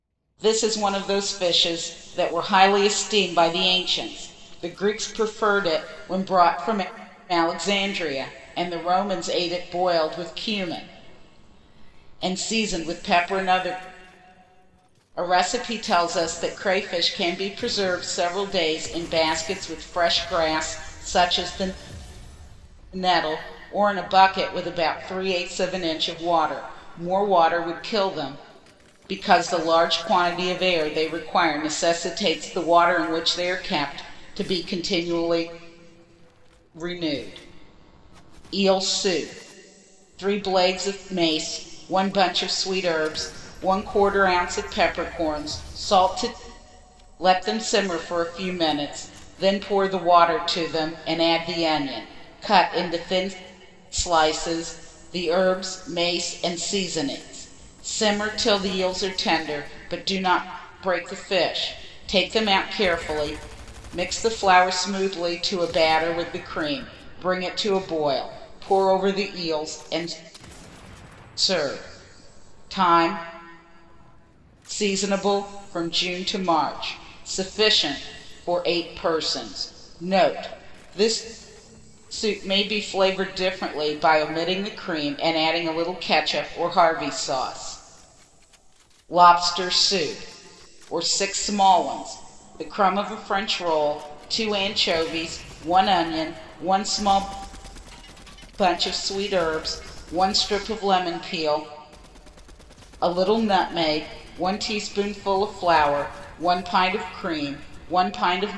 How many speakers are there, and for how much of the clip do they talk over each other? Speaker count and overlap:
one, no overlap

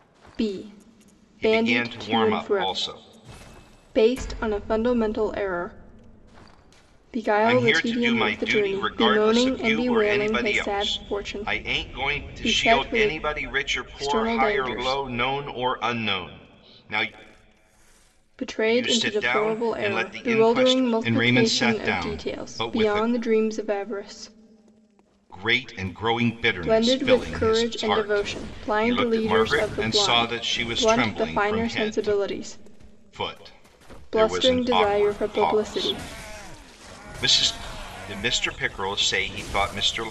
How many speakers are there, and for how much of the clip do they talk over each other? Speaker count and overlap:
two, about 49%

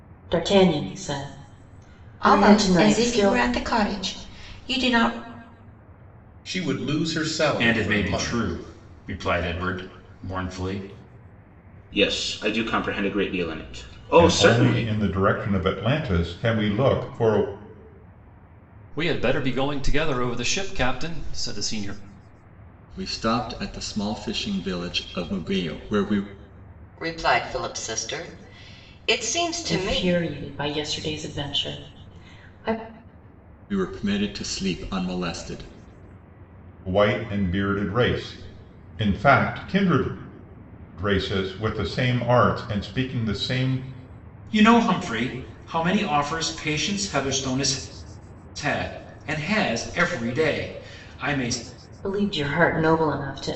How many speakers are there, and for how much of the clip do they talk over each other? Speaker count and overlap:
nine, about 6%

